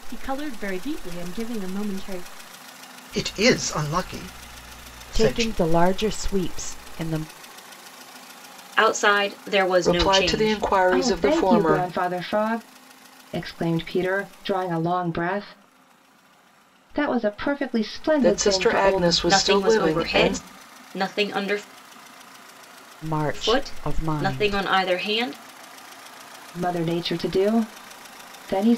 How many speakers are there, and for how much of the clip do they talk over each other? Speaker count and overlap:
six, about 20%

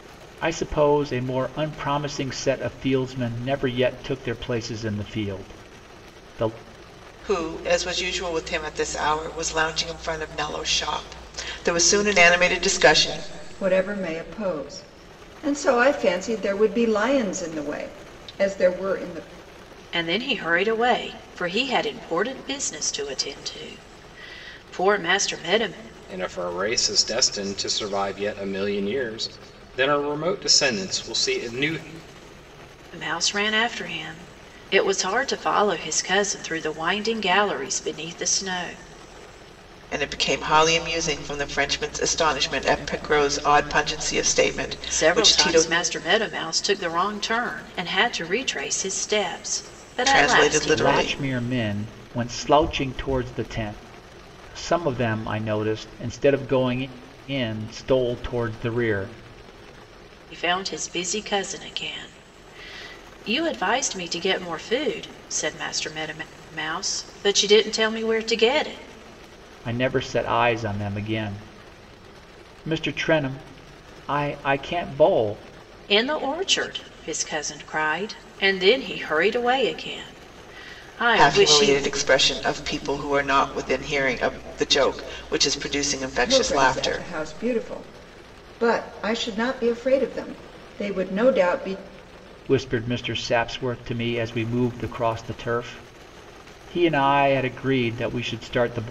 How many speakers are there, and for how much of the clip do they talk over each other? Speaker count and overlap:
five, about 4%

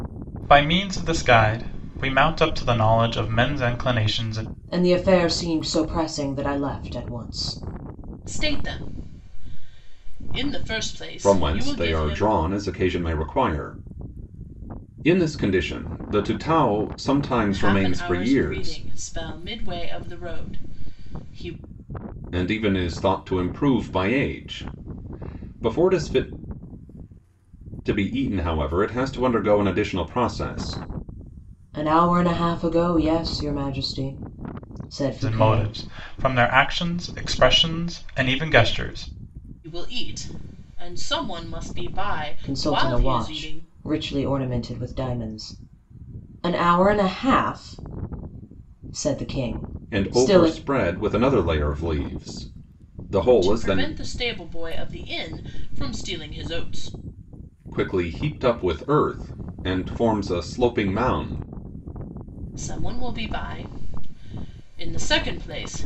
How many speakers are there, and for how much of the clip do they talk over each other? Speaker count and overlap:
four, about 8%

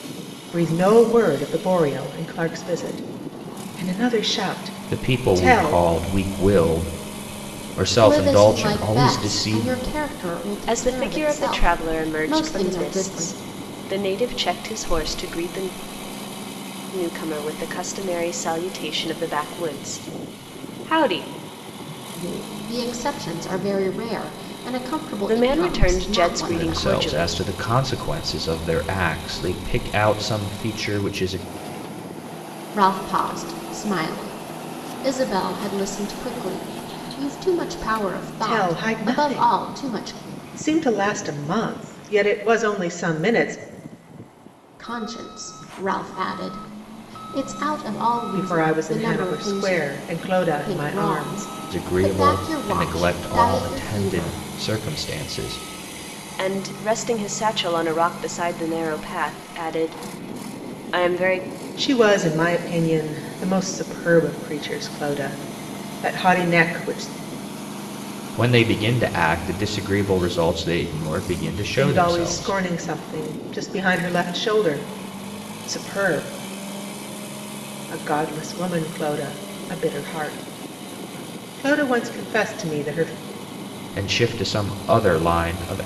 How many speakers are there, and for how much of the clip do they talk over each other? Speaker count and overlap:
four, about 18%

